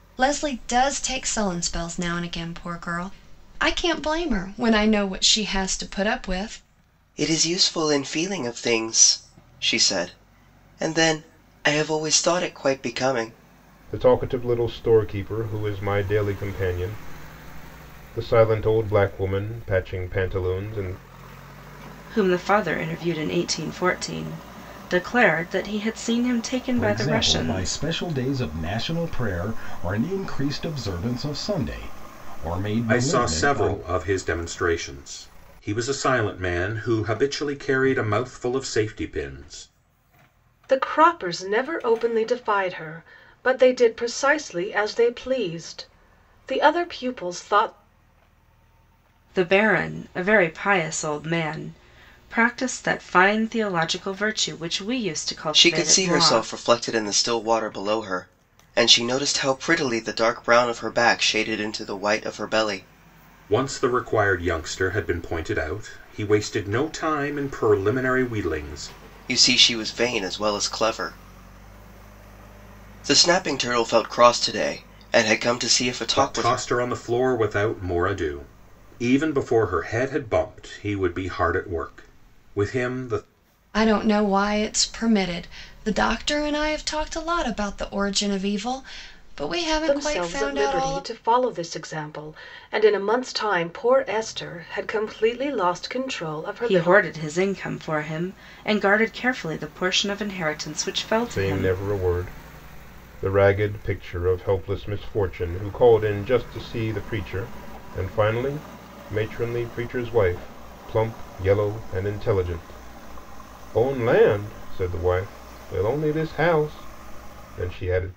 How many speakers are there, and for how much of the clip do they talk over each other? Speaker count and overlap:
7, about 5%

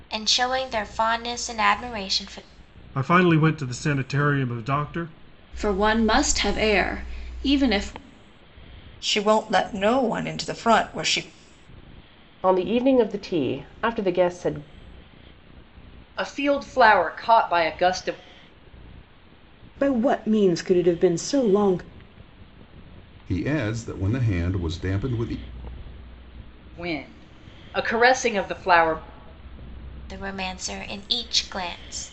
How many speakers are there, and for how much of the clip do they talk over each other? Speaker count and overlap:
8, no overlap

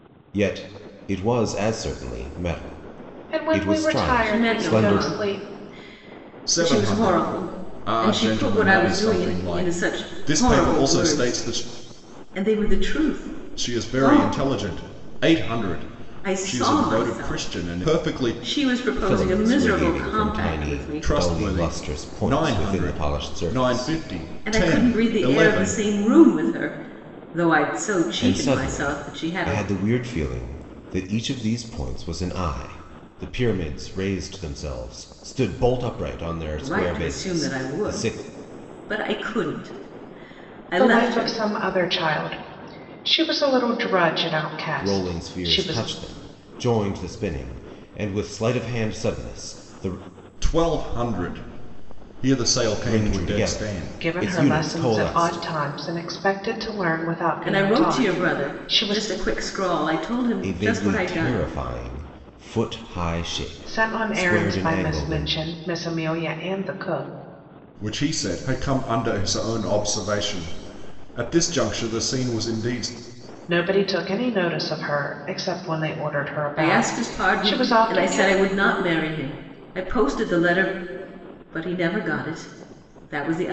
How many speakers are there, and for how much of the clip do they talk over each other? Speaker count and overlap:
4, about 36%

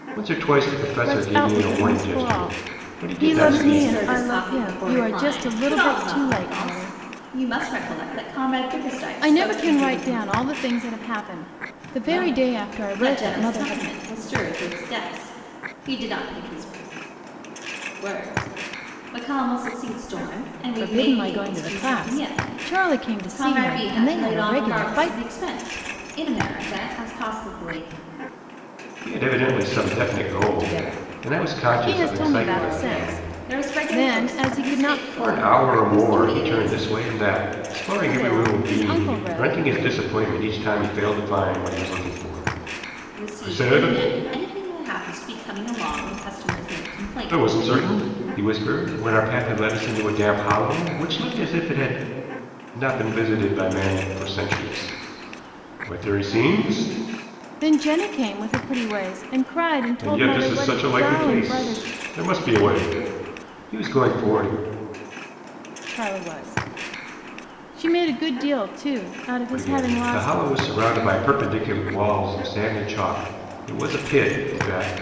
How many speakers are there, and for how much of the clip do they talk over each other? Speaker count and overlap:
3, about 33%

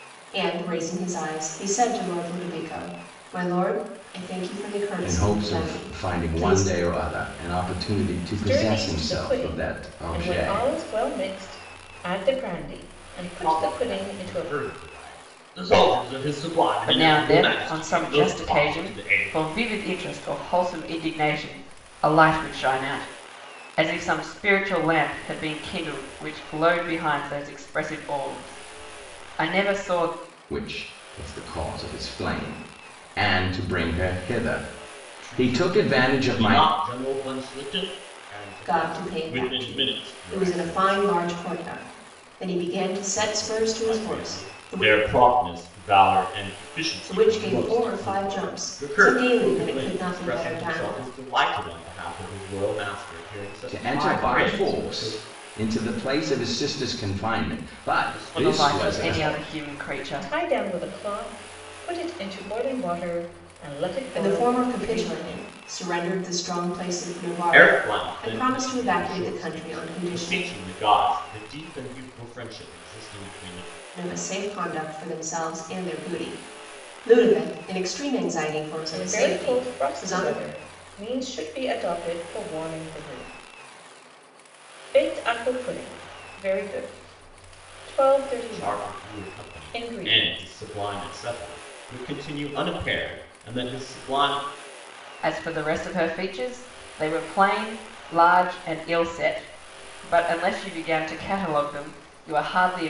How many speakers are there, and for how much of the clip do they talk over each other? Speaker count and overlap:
5, about 29%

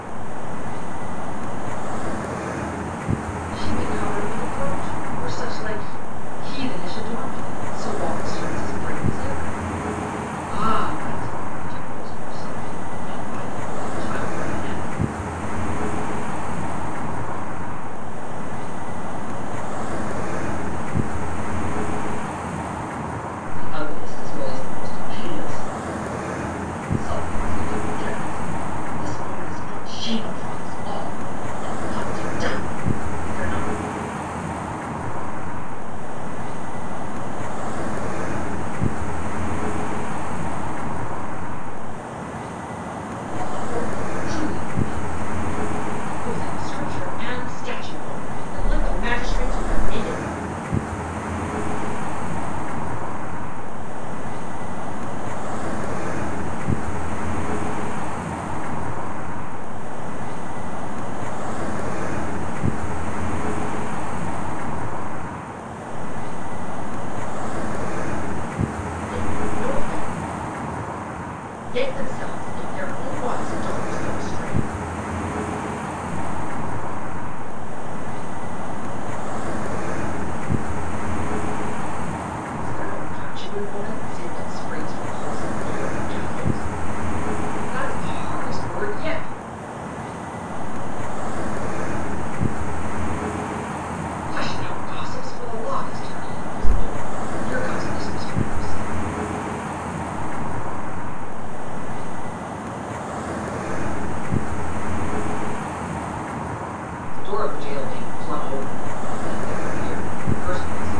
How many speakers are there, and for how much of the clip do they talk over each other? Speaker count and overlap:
2, no overlap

